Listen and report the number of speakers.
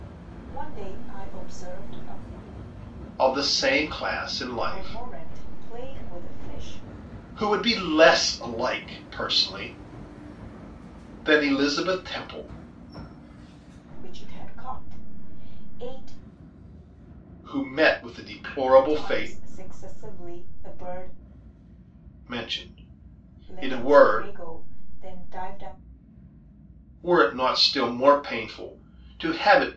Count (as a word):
two